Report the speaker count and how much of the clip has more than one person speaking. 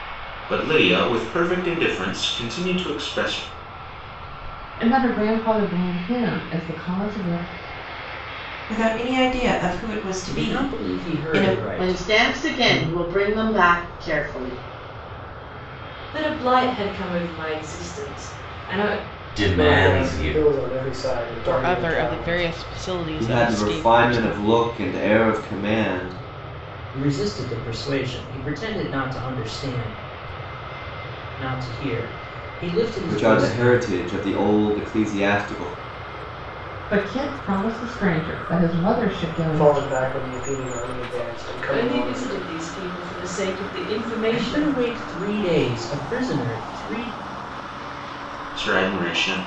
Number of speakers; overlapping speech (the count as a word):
ten, about 16%